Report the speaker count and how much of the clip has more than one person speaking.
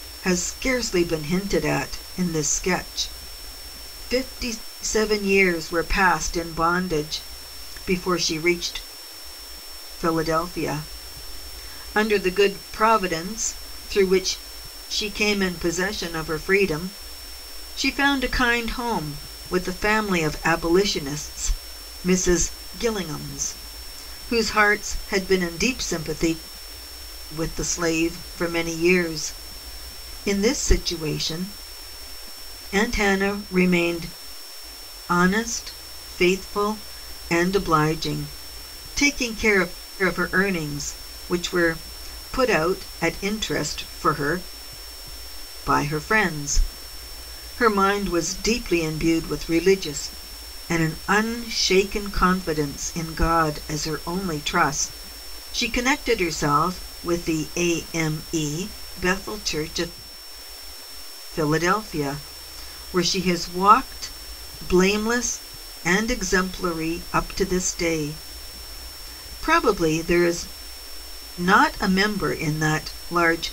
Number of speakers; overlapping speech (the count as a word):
one, no overlap